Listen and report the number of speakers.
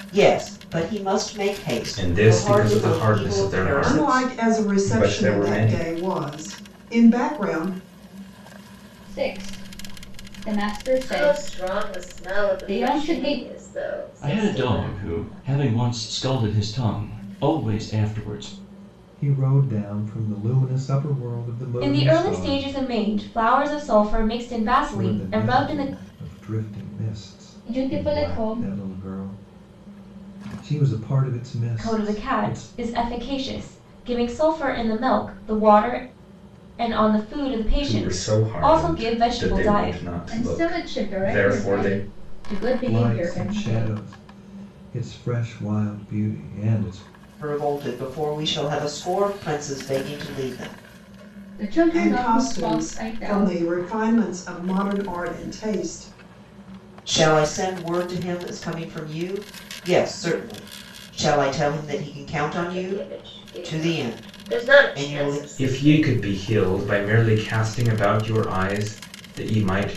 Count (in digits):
8